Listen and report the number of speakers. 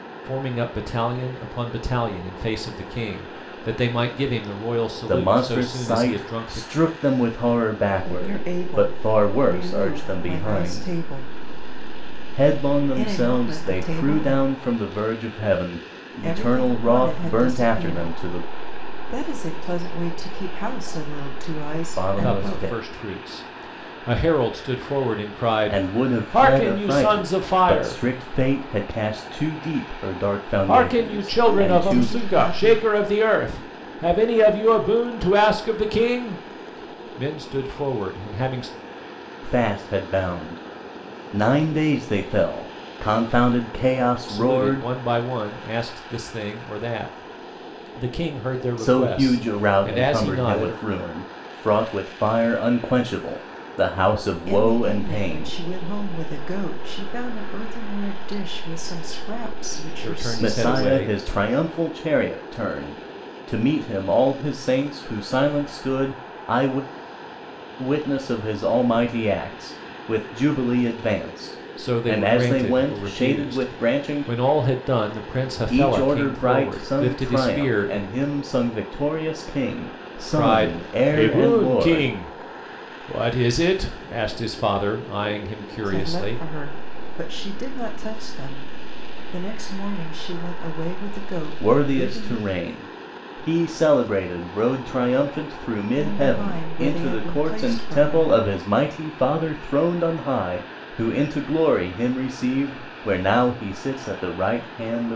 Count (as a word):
three